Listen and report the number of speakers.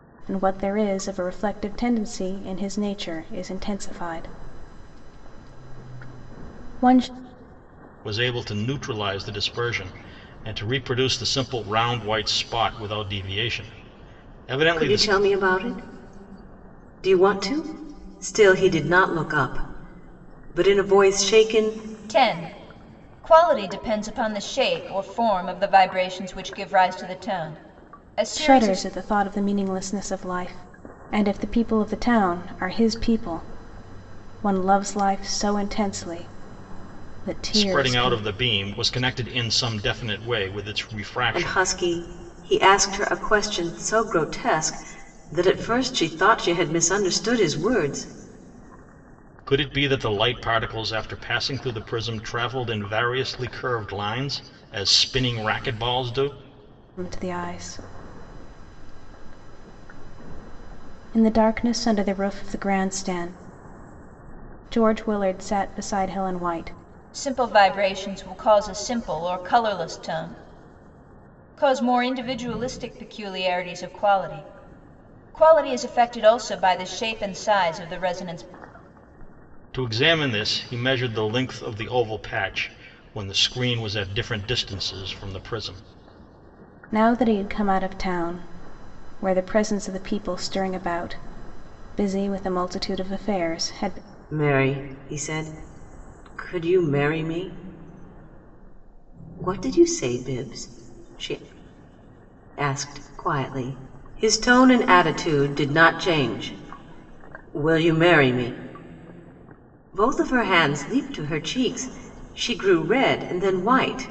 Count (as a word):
four